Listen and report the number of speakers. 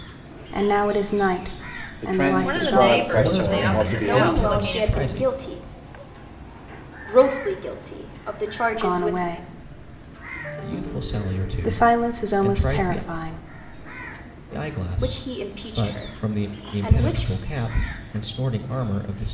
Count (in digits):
5